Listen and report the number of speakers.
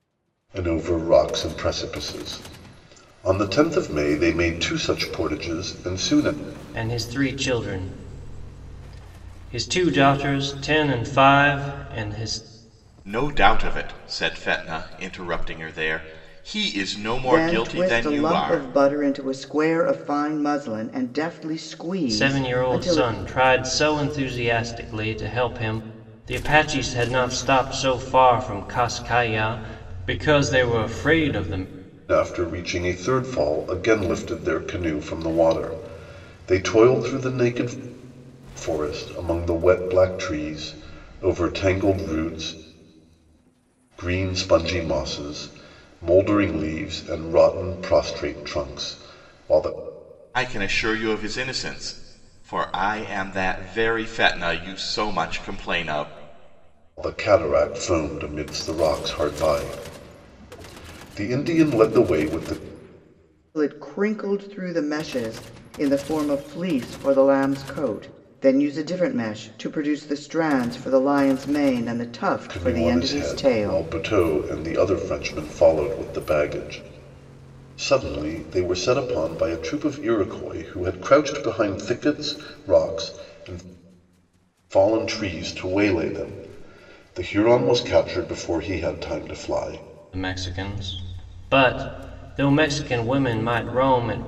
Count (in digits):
4